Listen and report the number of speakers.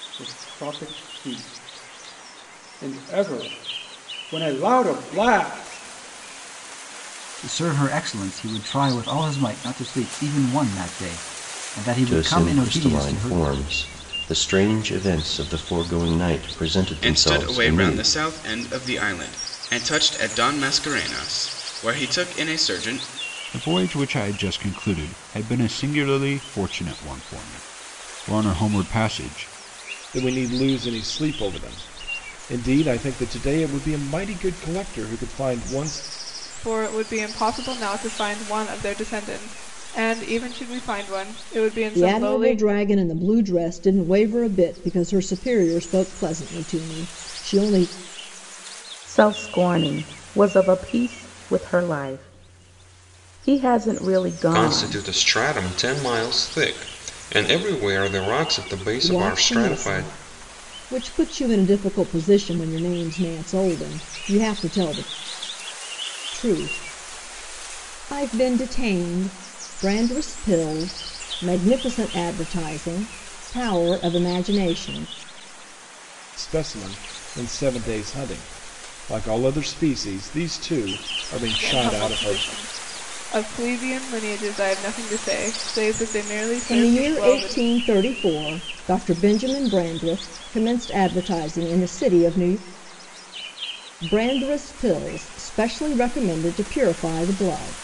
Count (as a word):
ten